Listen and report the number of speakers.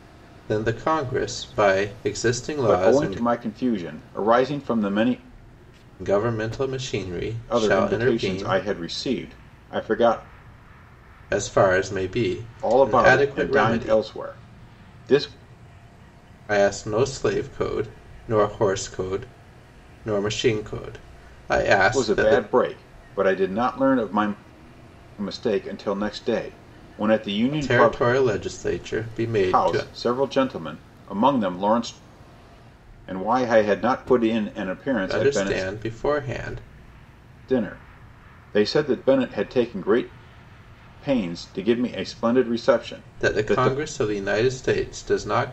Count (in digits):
2